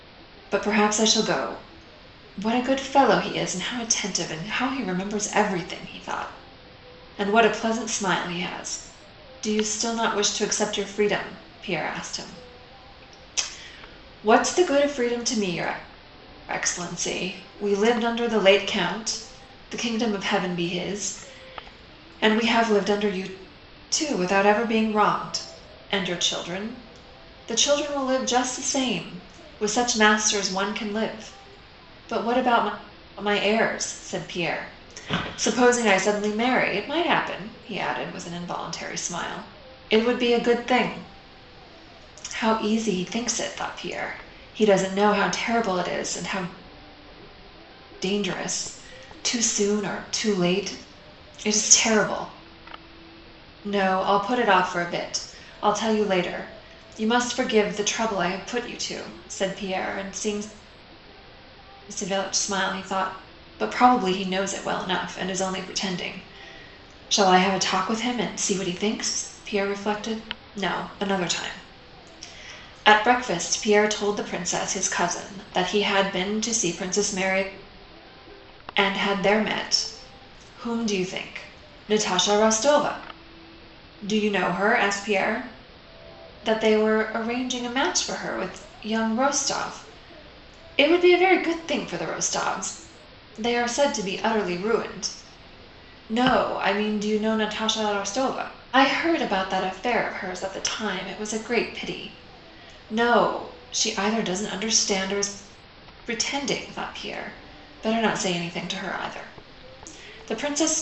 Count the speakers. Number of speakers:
1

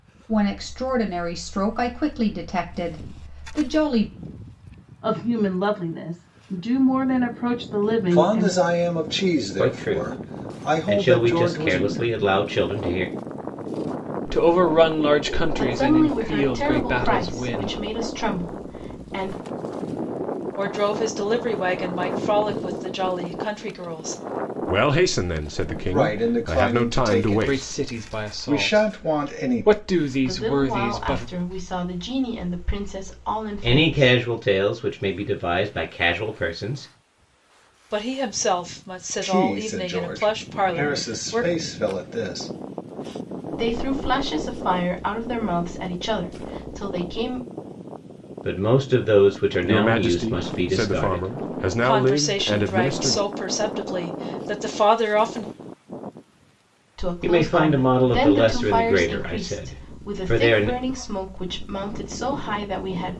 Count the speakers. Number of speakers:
8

